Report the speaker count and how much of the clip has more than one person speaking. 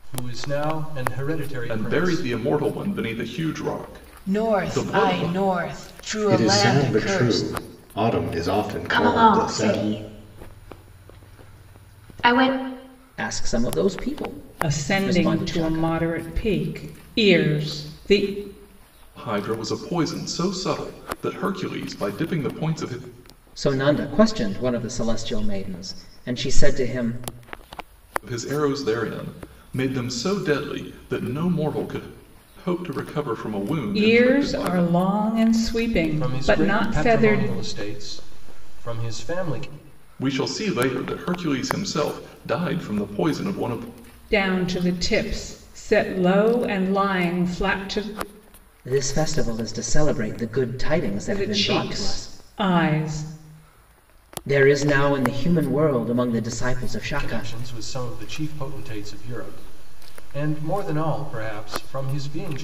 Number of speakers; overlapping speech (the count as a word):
seven, about 15%